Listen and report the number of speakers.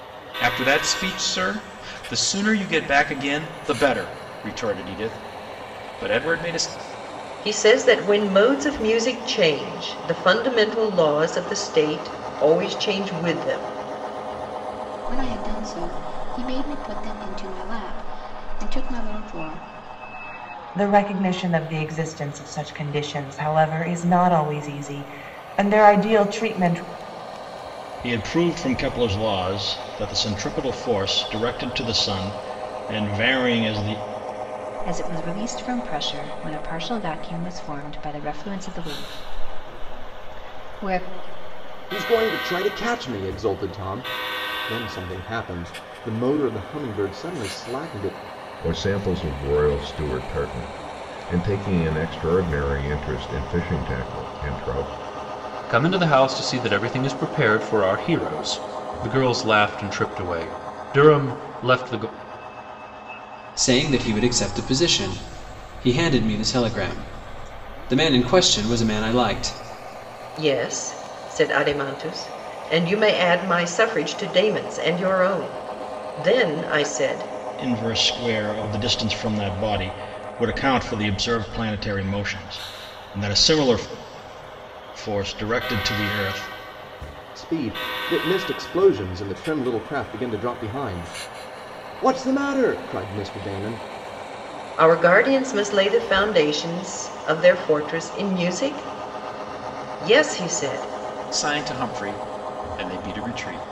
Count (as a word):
ten